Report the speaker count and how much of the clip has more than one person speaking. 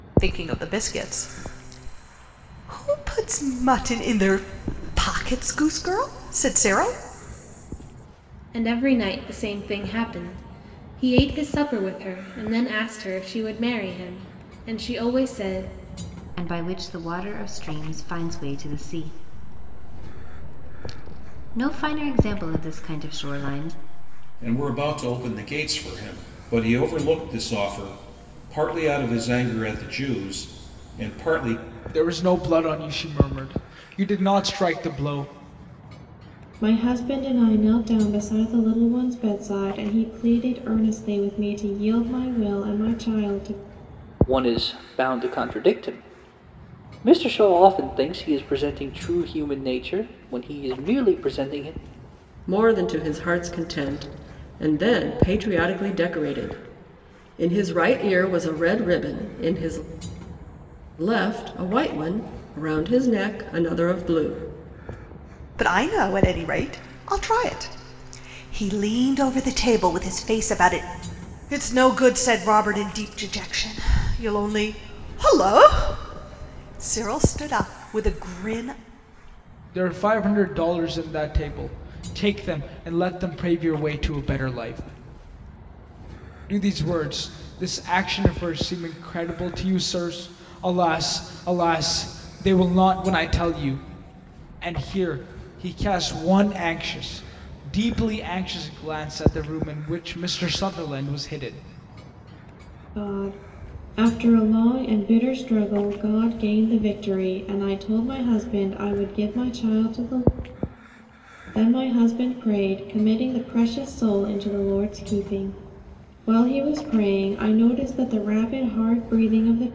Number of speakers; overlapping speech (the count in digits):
8, no overlap